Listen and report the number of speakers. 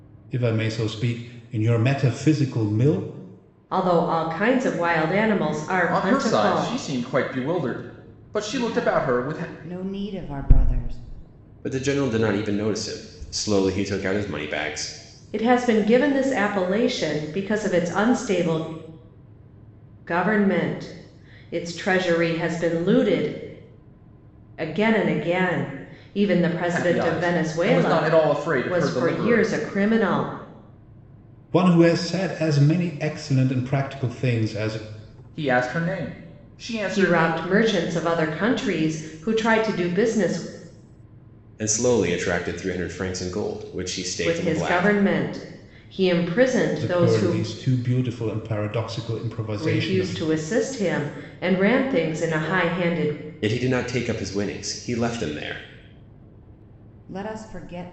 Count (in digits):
5